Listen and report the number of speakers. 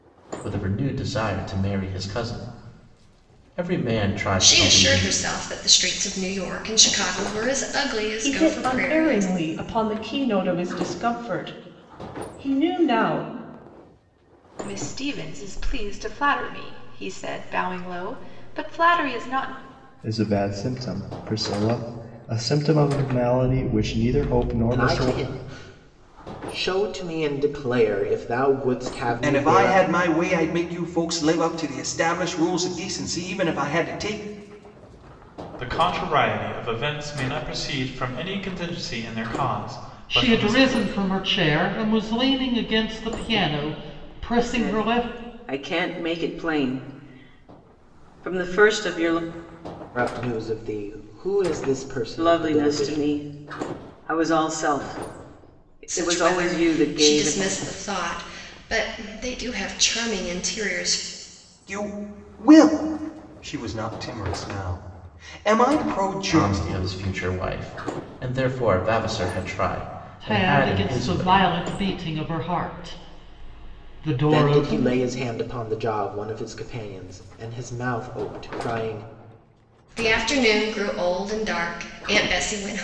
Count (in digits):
10